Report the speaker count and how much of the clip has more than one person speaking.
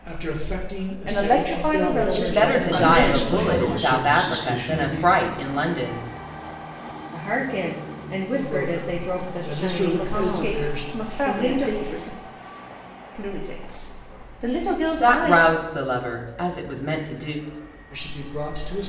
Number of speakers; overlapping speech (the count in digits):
5, about 42%